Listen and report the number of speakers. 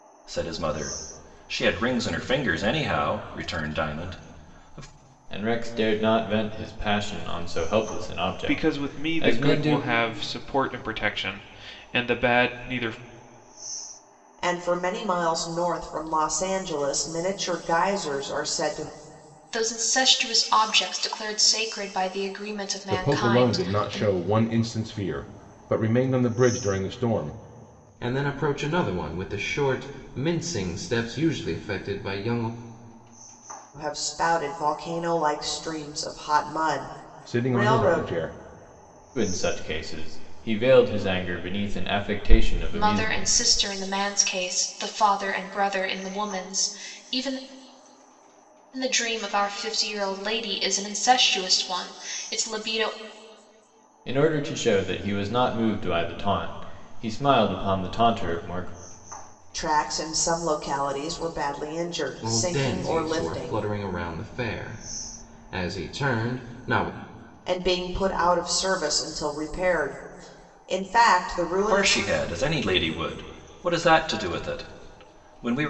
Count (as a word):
seven